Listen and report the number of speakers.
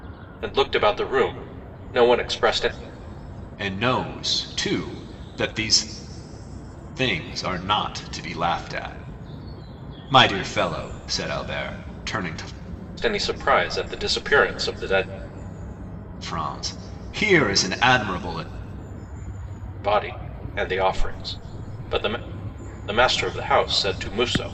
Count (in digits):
2